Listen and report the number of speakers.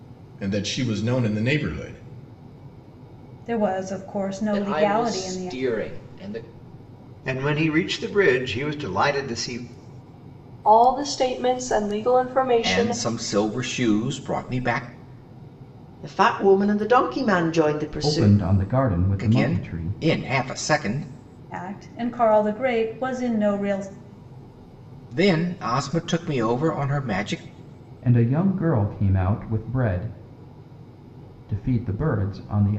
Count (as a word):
eight